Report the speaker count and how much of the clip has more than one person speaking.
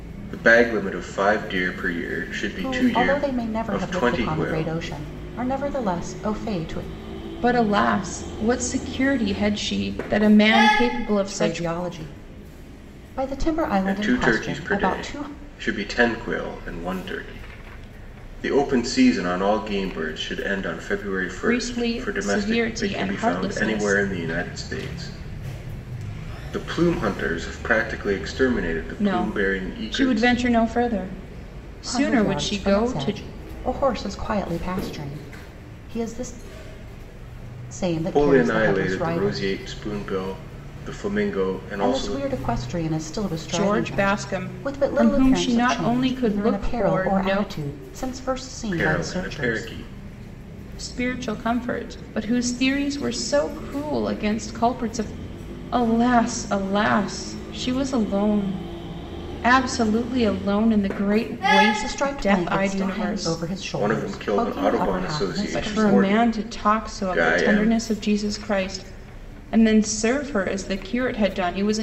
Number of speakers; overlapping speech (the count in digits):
3, about 31%